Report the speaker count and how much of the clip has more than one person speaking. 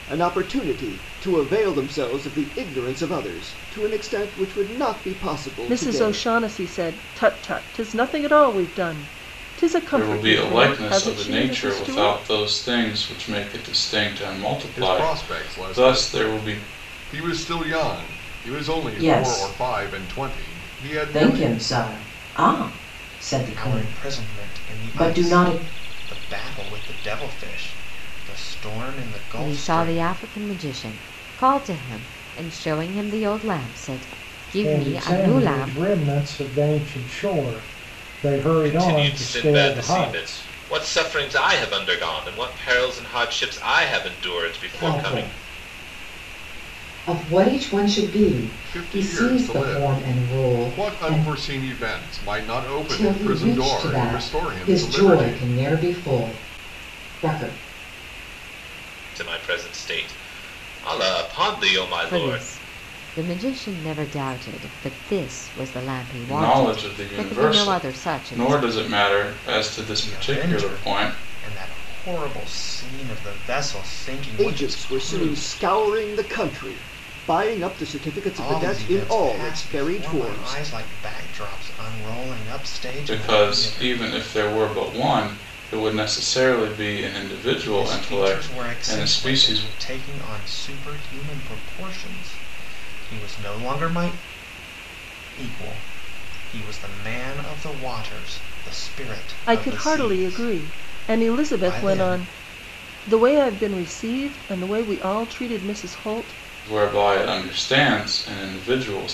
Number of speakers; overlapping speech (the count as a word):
ten, about 30%